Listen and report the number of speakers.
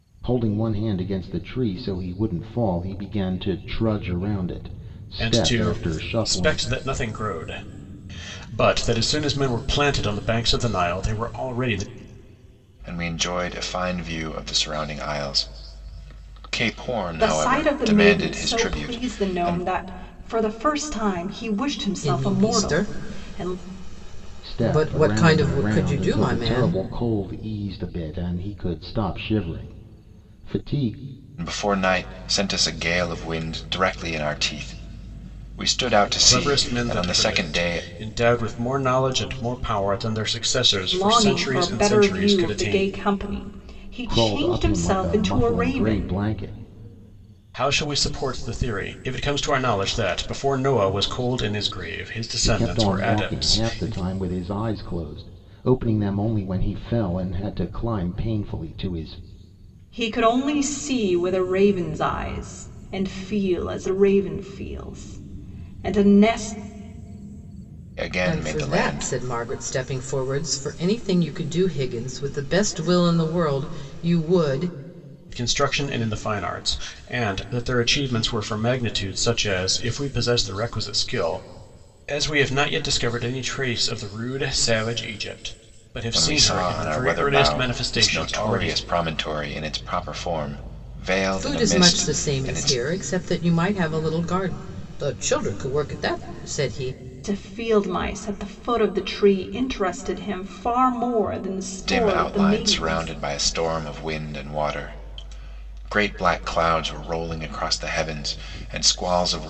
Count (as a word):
five